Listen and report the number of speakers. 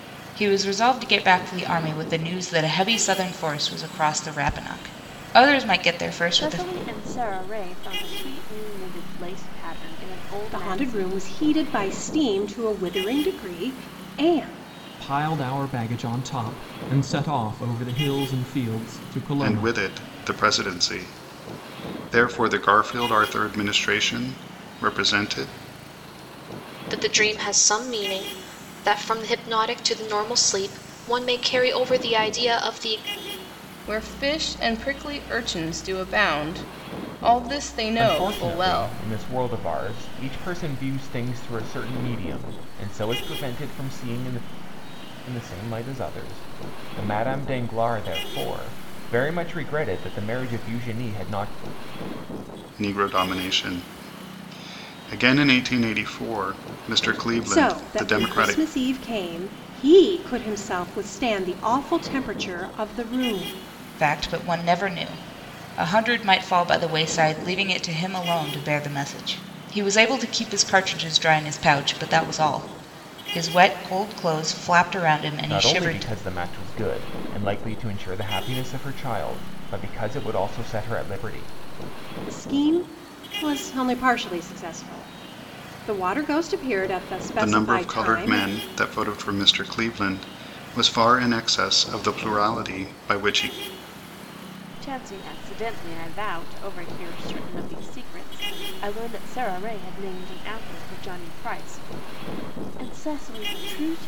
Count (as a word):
eight